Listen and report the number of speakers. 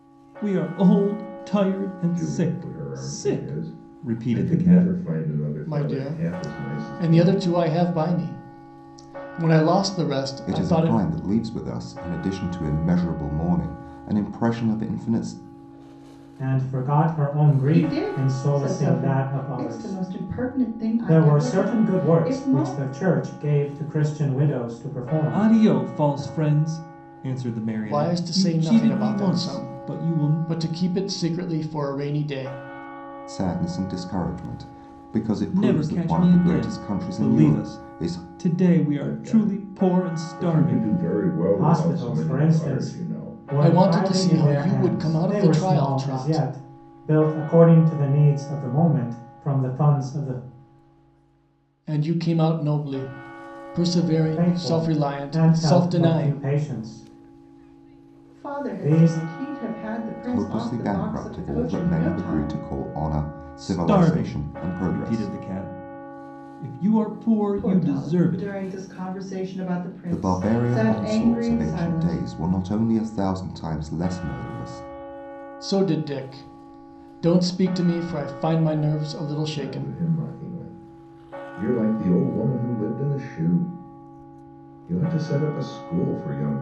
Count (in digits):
6